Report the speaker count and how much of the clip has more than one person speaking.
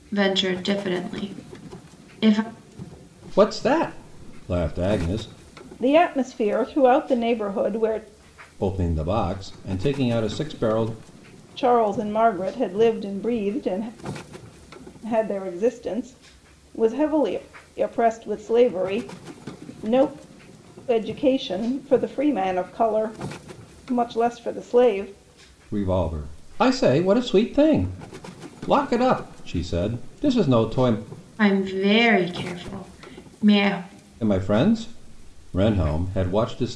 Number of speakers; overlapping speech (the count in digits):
3, no overlap